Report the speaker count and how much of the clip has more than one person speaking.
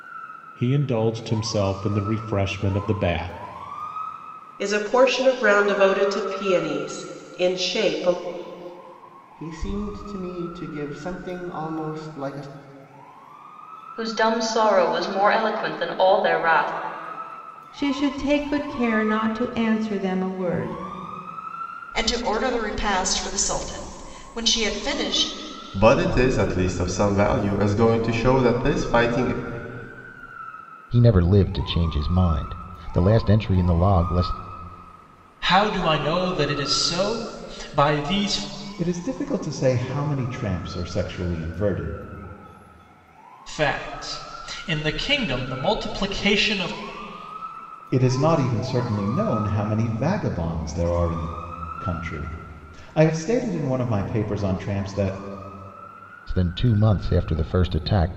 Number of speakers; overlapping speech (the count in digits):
10, no overlap